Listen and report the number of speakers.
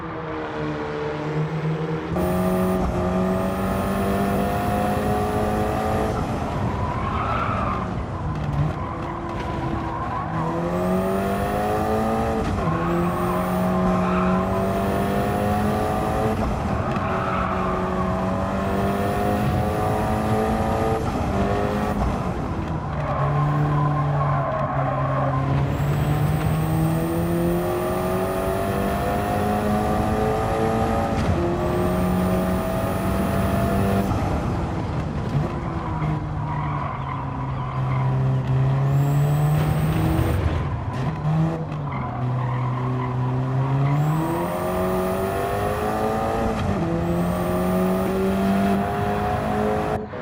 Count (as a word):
zero